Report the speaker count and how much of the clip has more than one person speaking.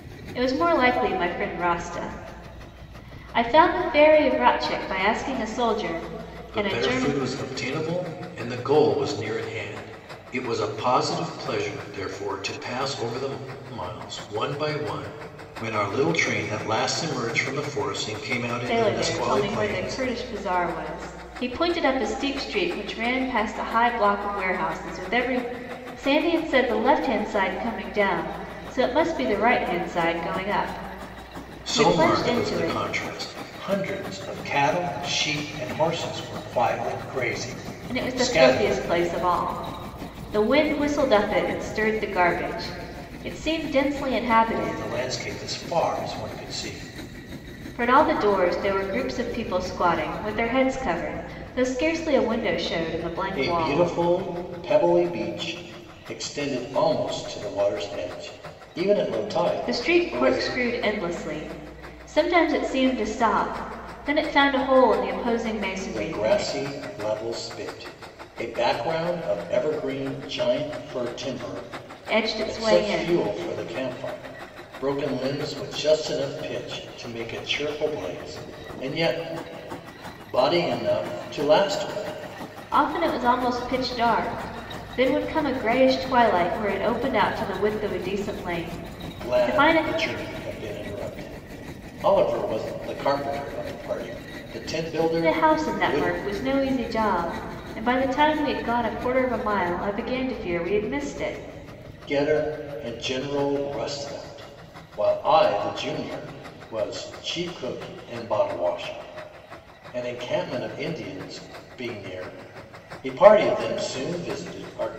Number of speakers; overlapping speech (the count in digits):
2, about 8%